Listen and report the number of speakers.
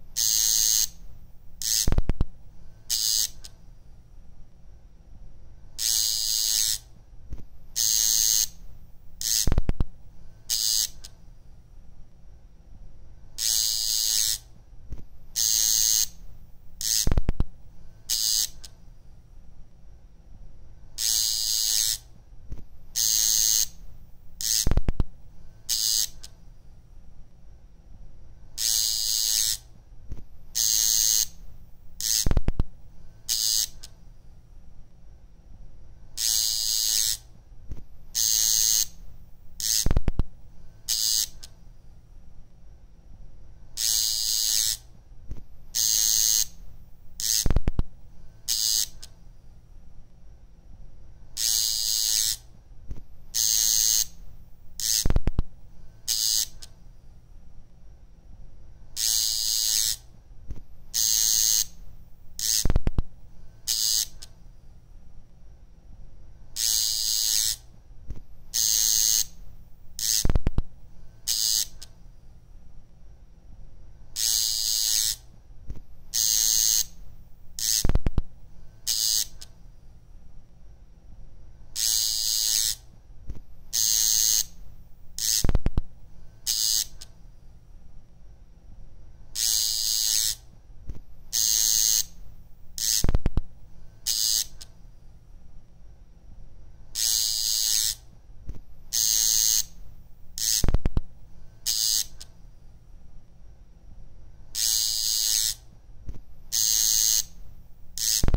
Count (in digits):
0